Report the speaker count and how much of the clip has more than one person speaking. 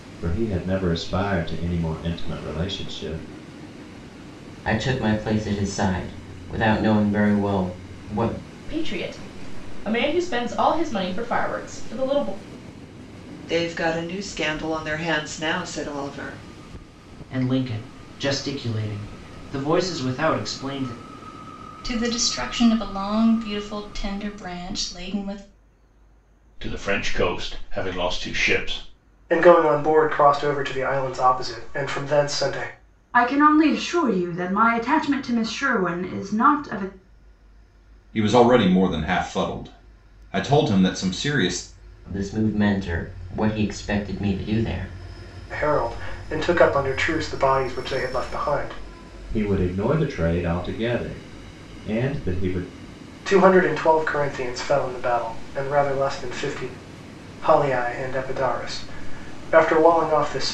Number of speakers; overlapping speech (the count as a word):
ten, no overlap